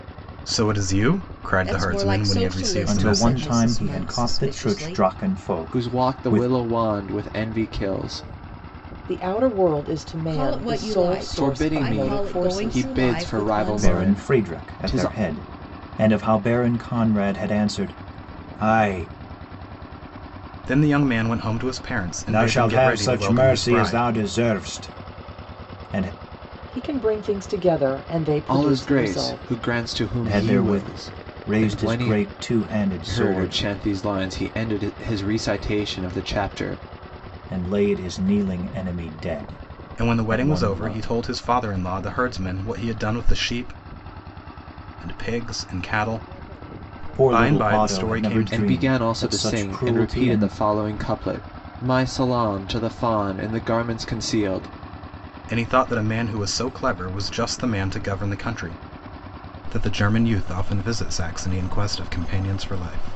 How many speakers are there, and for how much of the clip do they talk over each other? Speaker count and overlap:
5, about 31%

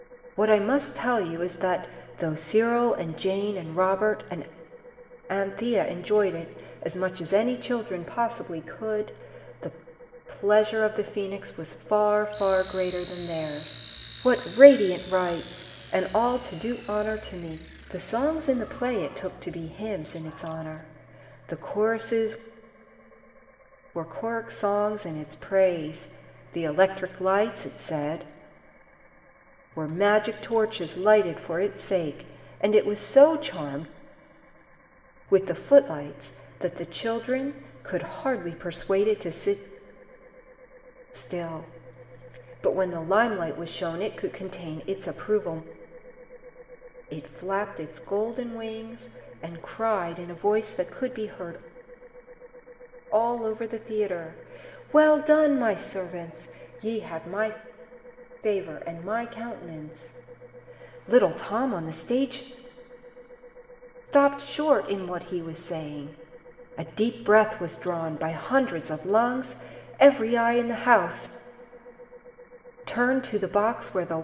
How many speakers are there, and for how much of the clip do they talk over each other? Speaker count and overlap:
1, no overlap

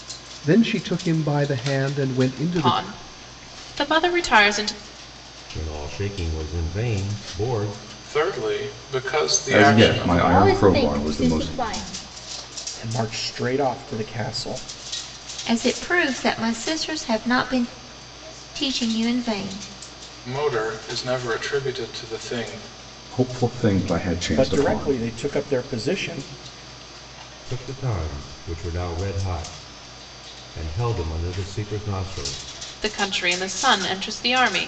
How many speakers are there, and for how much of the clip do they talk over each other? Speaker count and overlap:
8, about 9%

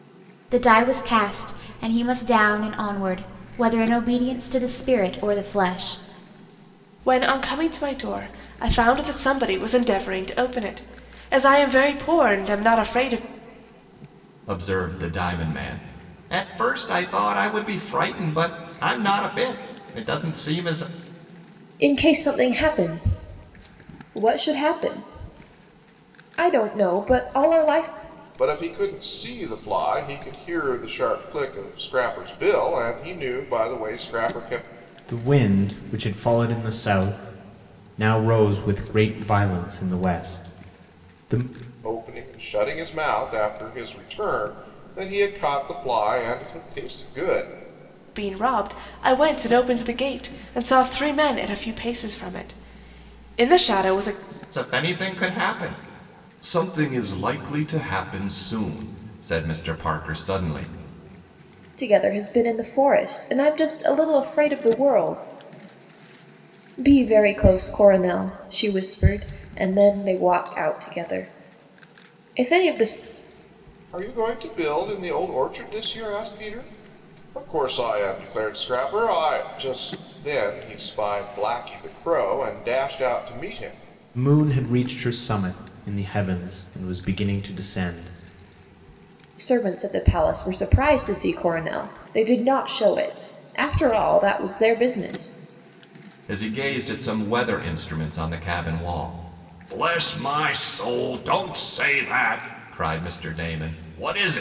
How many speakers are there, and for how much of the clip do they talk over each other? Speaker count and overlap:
6, no overlap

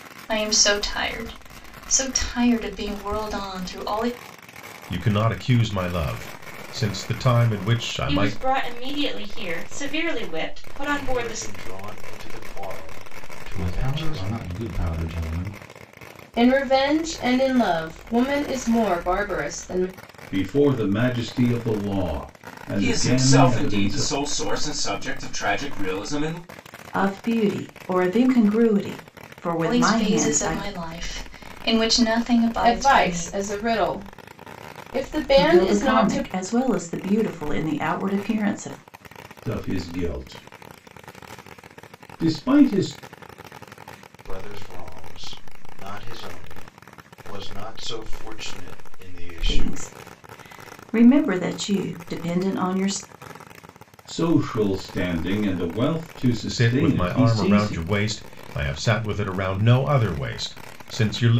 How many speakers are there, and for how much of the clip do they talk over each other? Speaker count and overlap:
9, about 12%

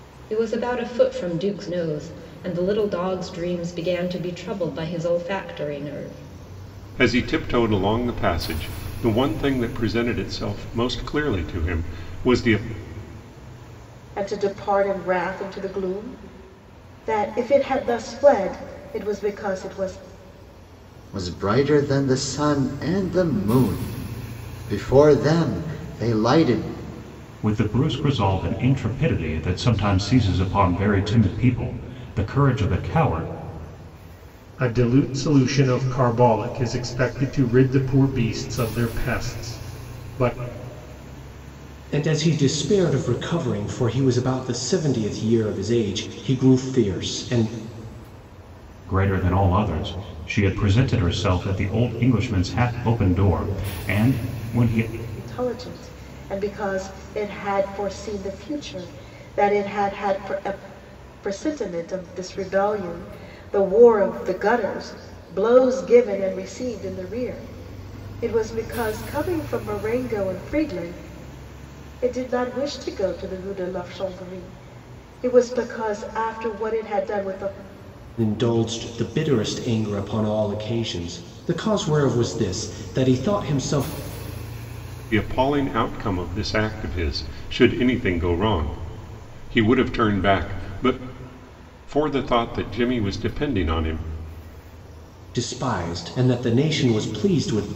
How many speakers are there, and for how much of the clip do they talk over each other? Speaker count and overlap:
7, no overlap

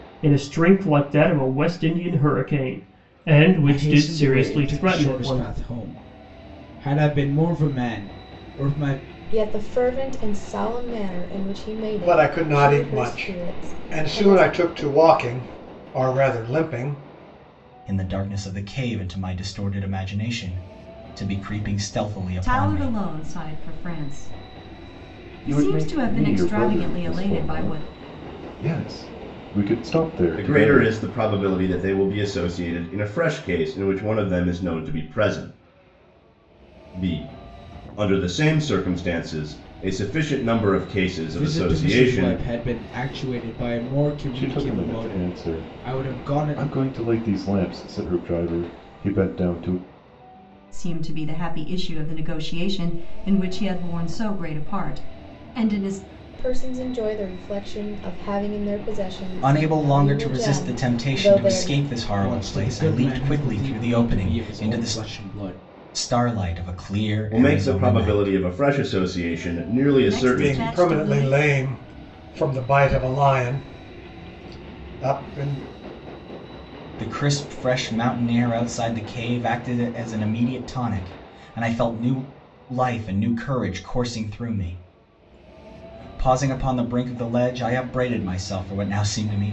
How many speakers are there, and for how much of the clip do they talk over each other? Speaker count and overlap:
8, about 21%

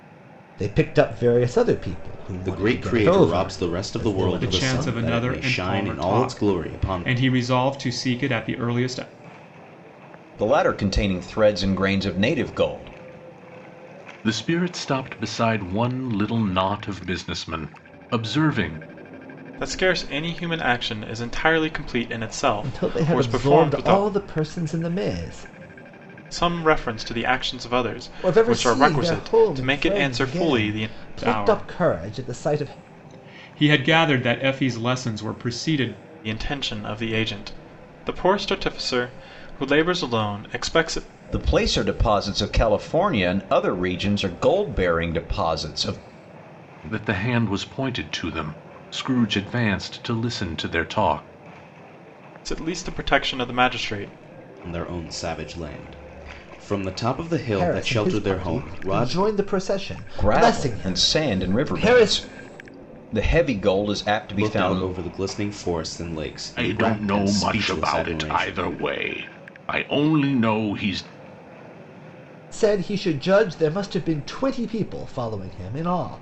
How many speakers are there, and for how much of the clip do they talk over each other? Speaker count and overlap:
6, about 22%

